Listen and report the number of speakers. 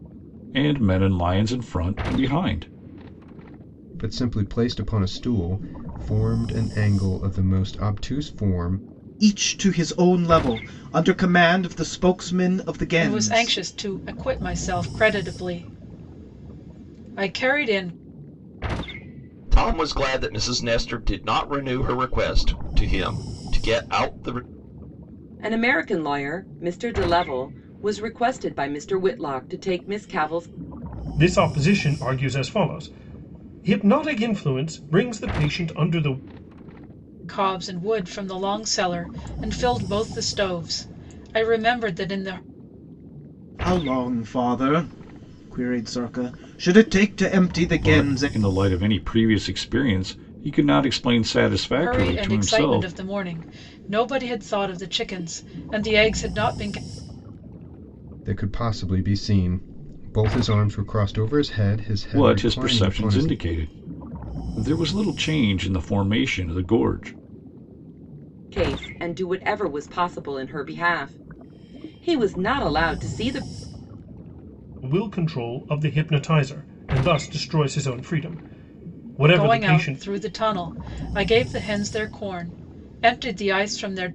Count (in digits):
7